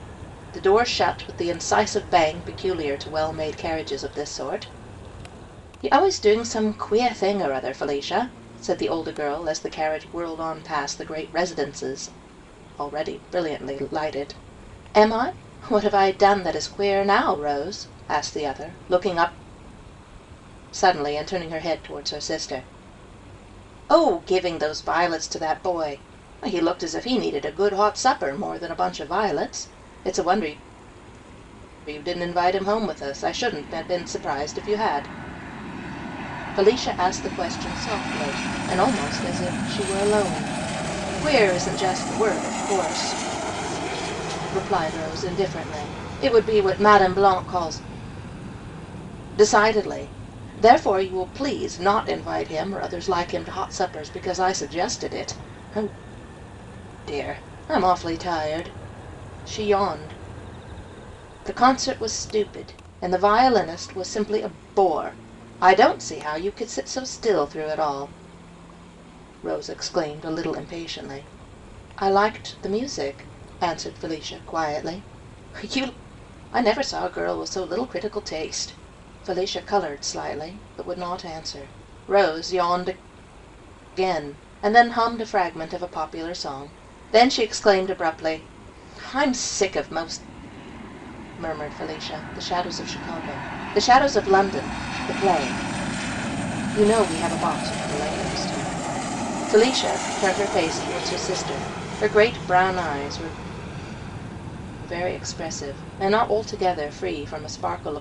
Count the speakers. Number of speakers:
one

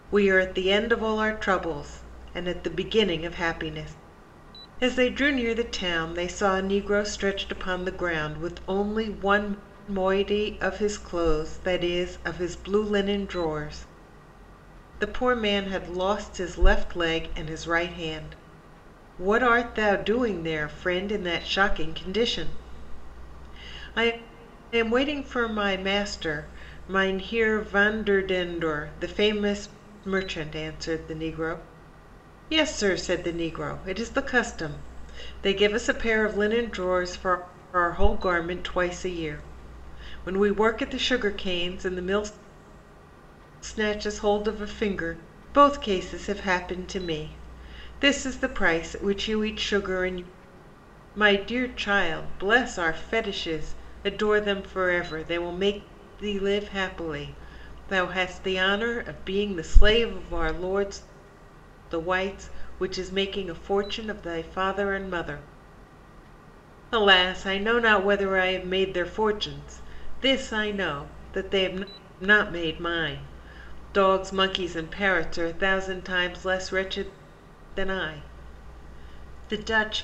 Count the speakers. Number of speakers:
one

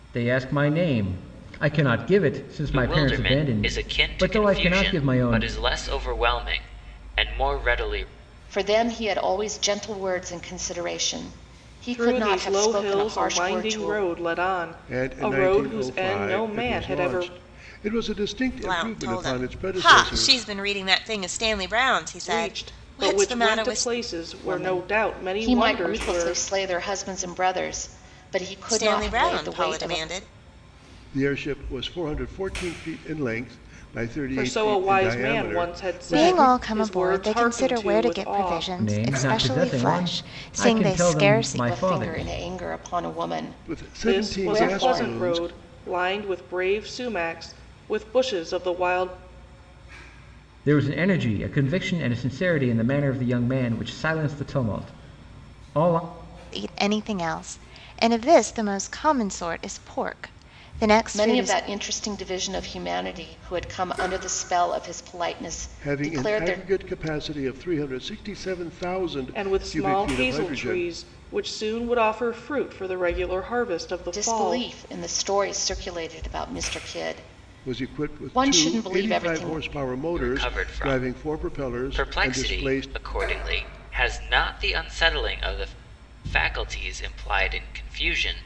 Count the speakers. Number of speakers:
six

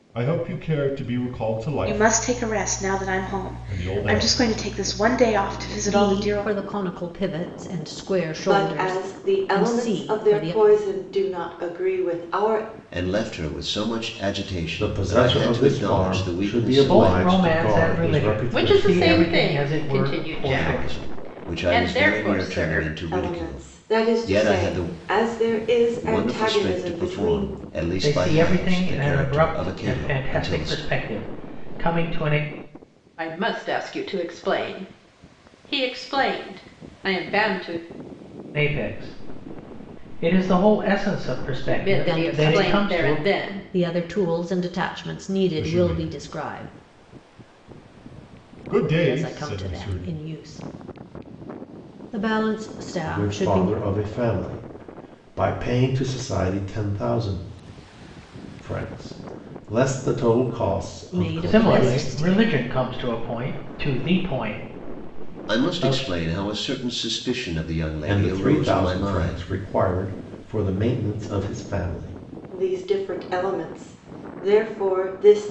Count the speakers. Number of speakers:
eight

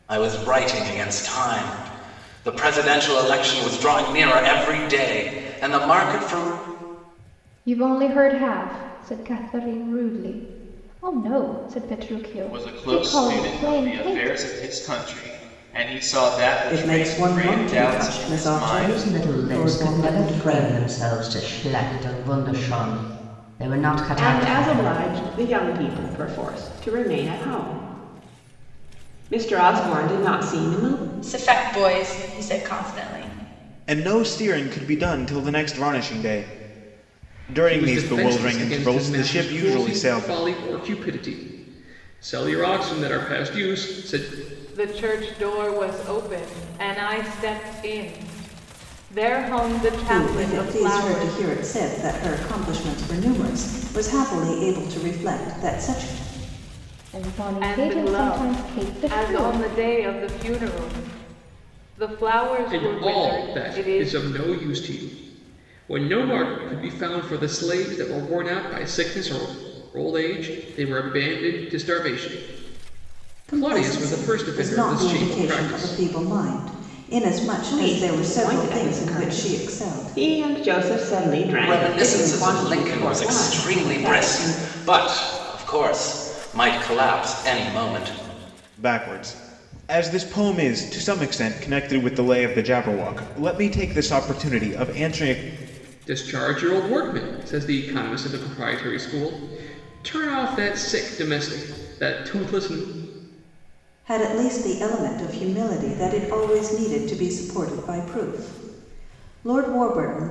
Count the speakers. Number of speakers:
ten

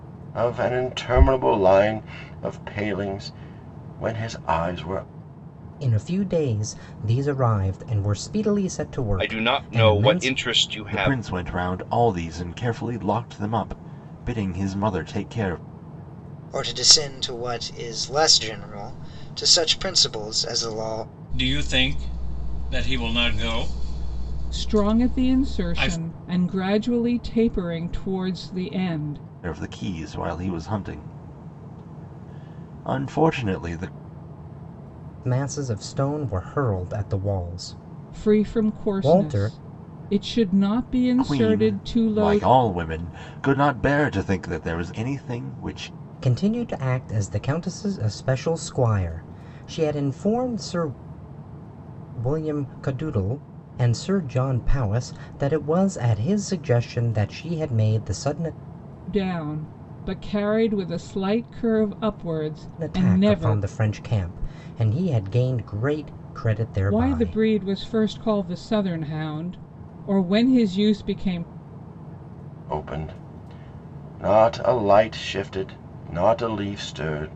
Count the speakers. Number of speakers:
seven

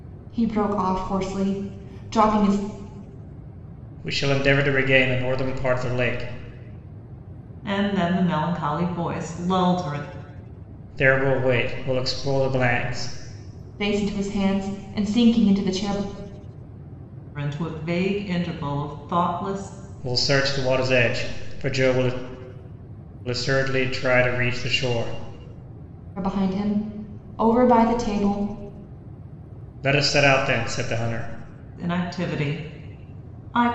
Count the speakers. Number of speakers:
three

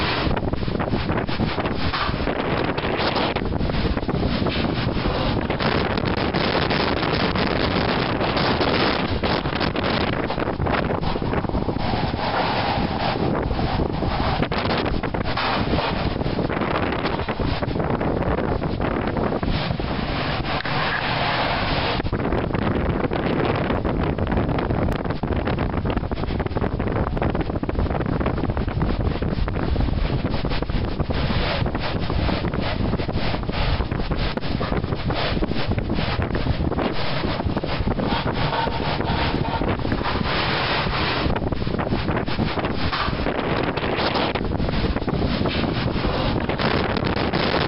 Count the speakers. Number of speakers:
zero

